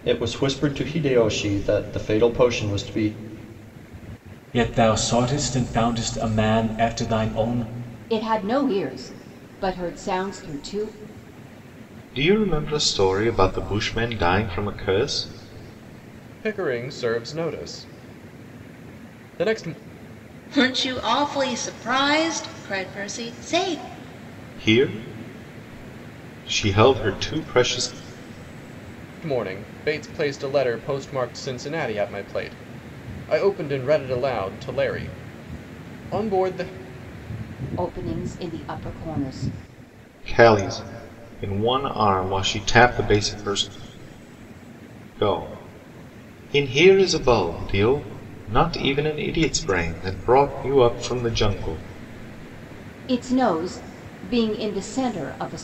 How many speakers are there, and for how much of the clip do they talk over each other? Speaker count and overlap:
6, no overlap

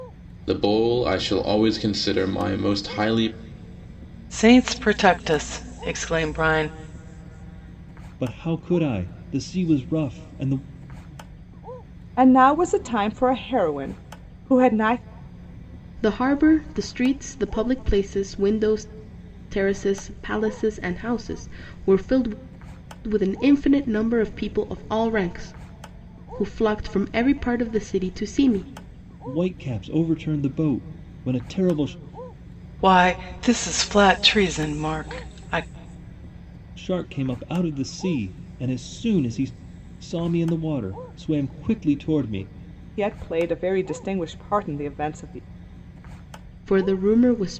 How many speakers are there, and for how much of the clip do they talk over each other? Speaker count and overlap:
5, no overlap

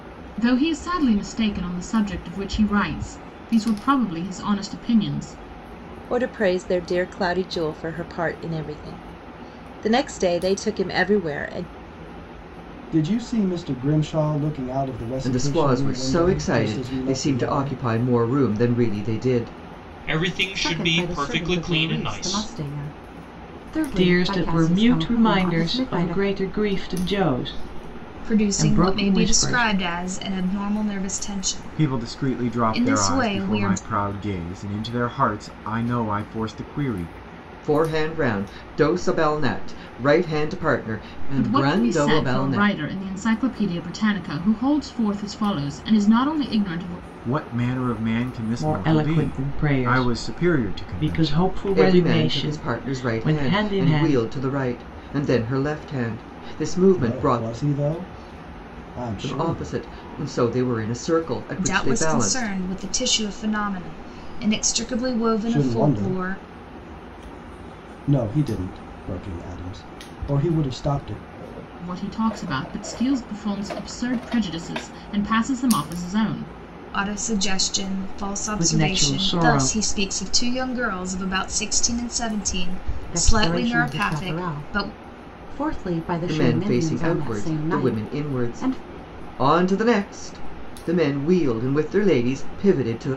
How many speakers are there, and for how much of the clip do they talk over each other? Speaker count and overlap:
9, about 28%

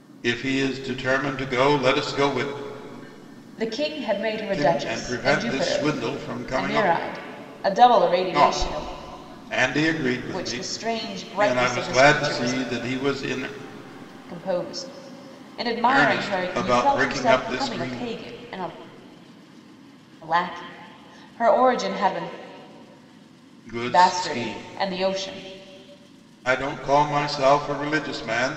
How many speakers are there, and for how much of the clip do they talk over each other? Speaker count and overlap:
2, about 24%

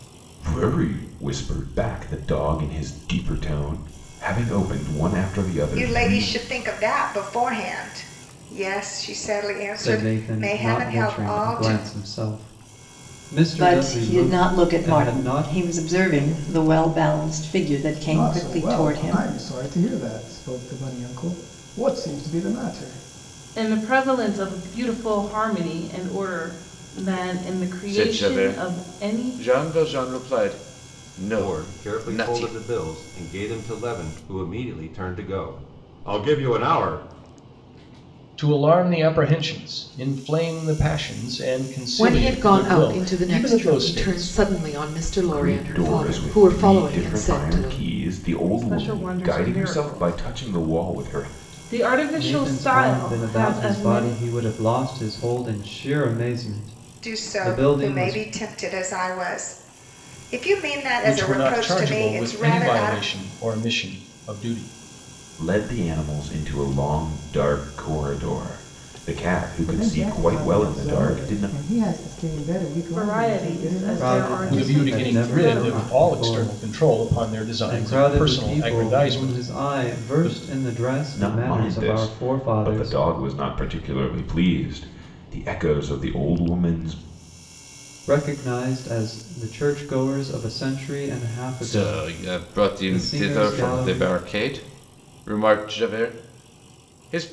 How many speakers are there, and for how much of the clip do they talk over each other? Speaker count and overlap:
10, about 36%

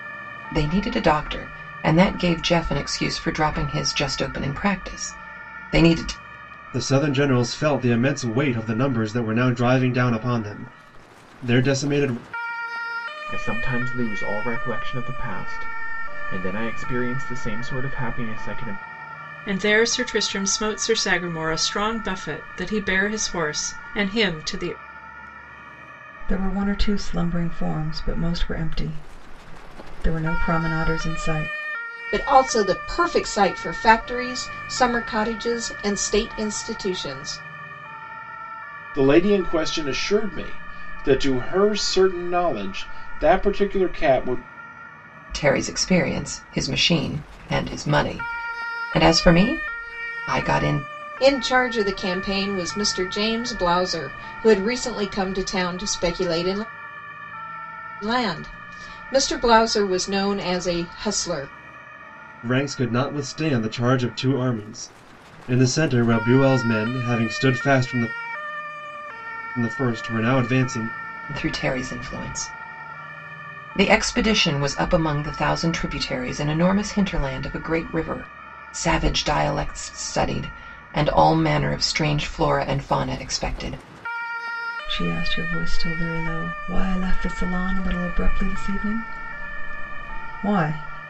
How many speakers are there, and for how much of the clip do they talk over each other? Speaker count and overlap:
7, no overlap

